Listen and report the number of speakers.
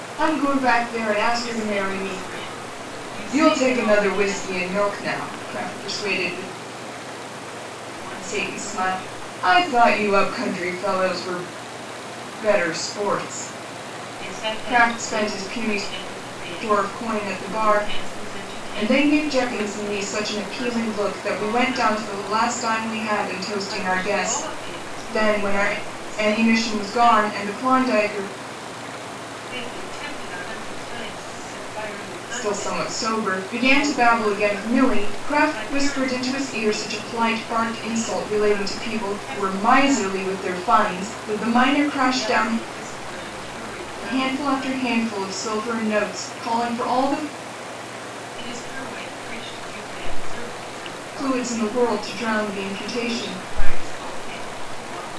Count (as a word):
two